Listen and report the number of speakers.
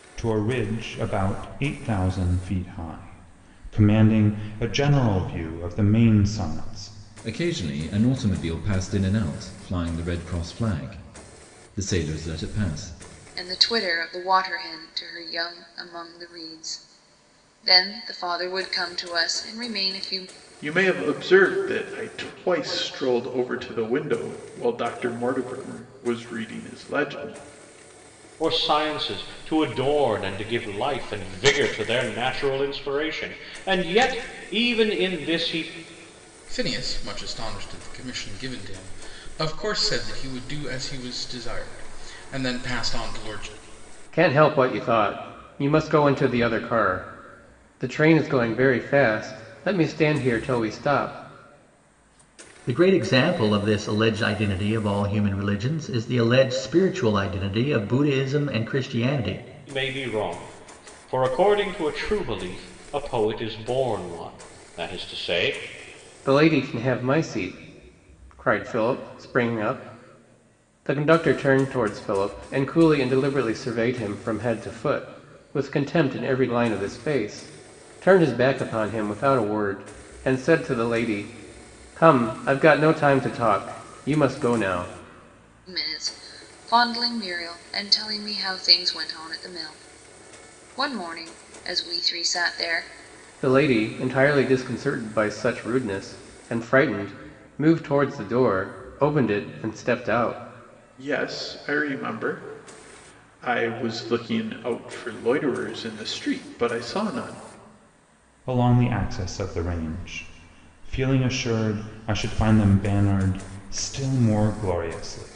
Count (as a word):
eight